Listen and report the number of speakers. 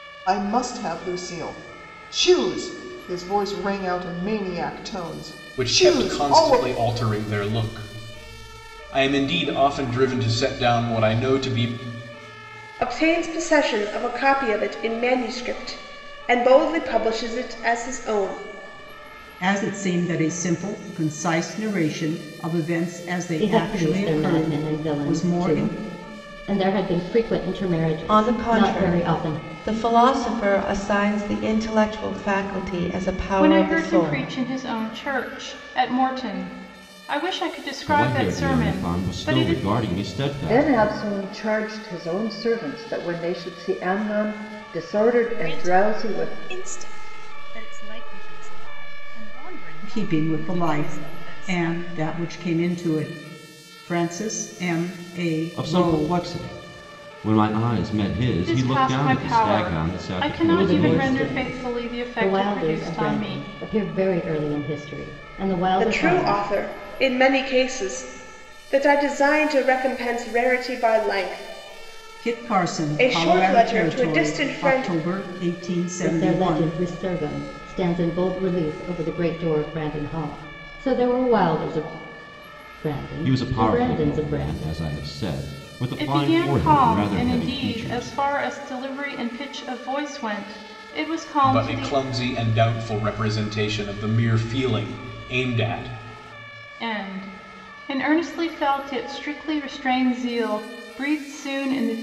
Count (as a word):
ten